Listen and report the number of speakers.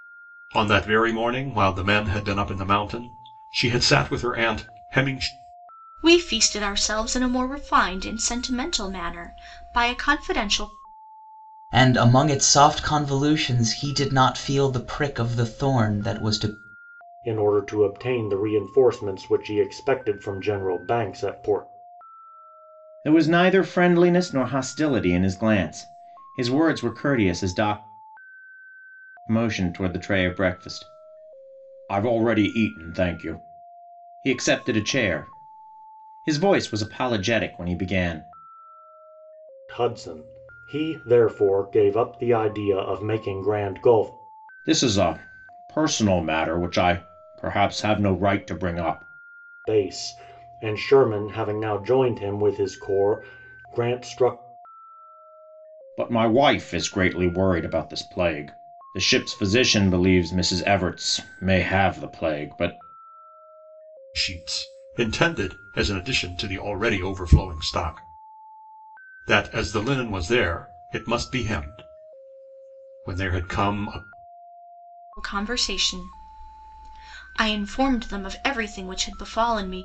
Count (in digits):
5